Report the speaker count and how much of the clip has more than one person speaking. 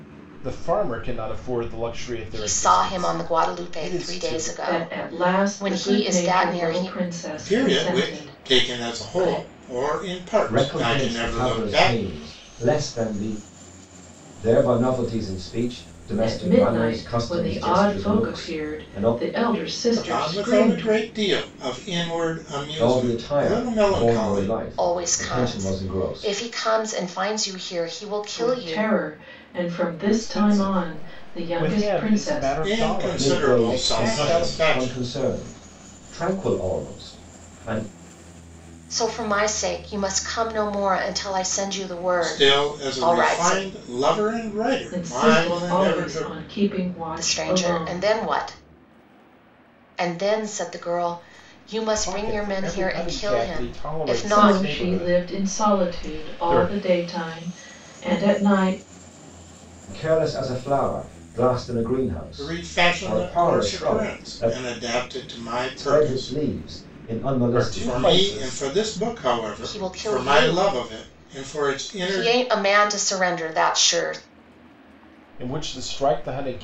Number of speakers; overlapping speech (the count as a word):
five, about 47%